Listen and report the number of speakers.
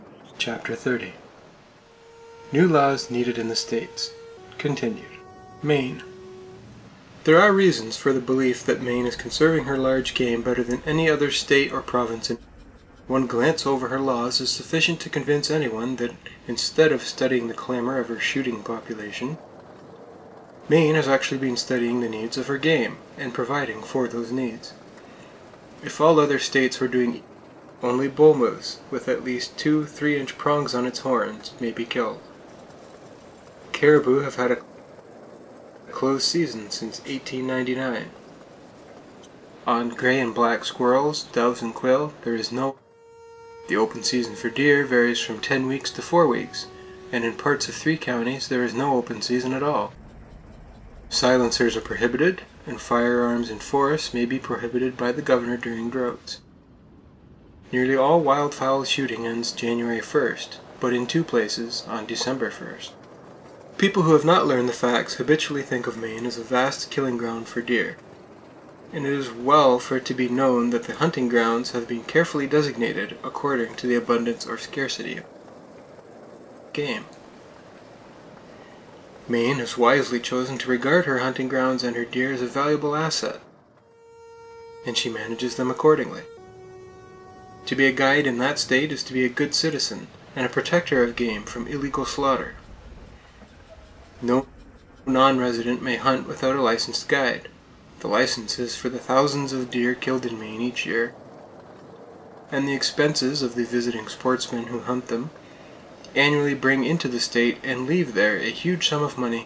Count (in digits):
1